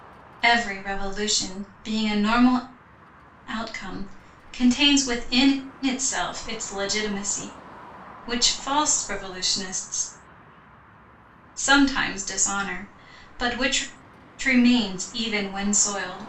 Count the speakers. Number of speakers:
one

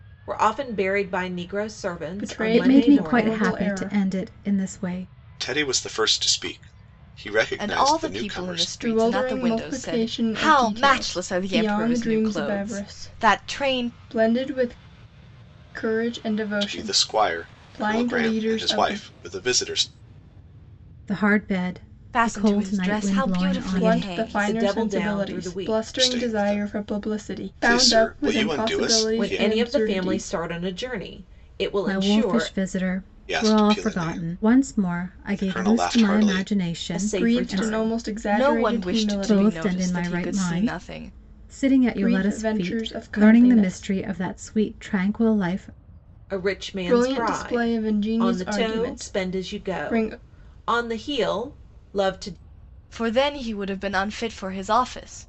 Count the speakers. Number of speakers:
five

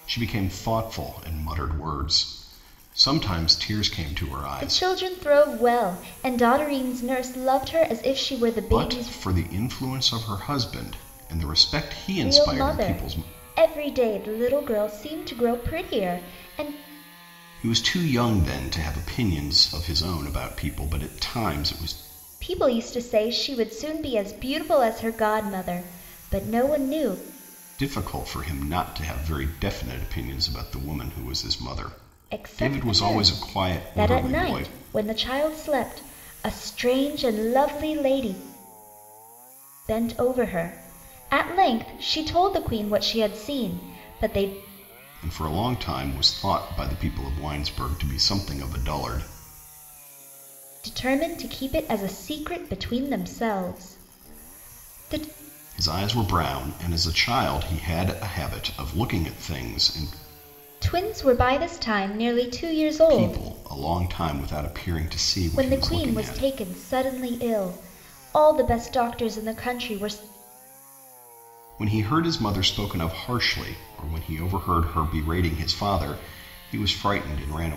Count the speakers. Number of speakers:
two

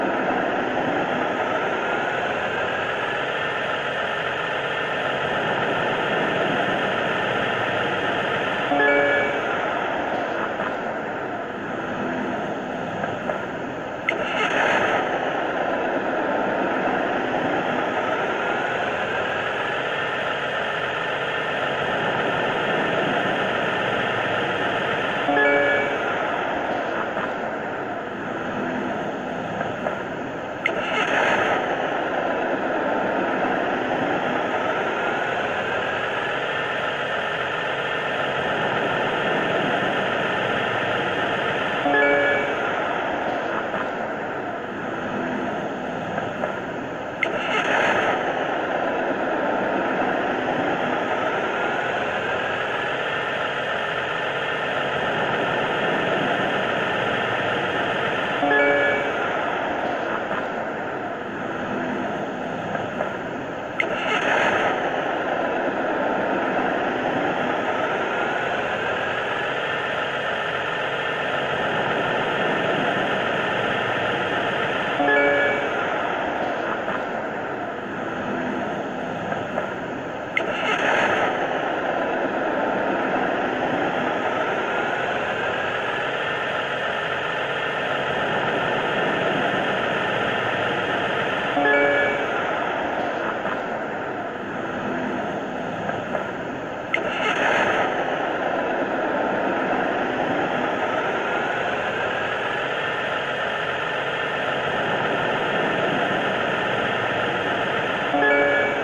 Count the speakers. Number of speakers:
zero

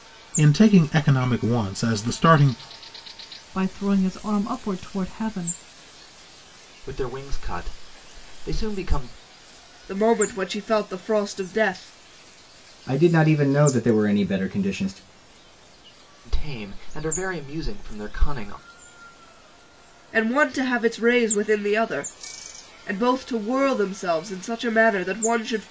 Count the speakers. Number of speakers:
five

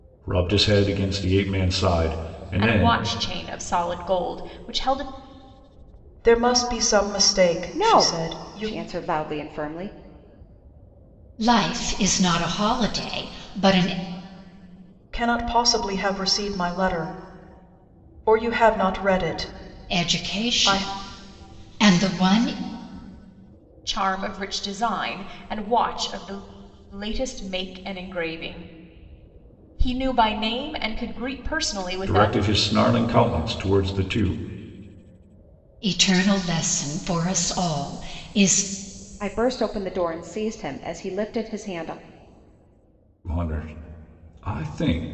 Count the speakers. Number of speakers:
five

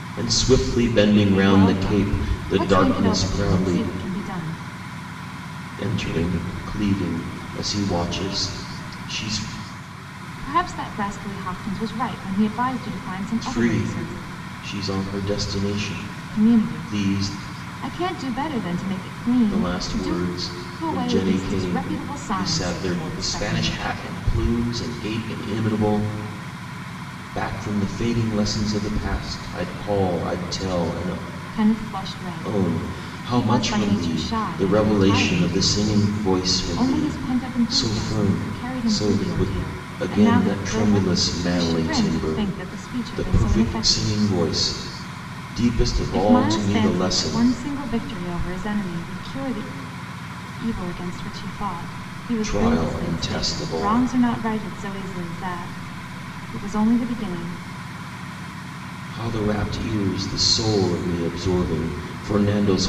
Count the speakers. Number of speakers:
two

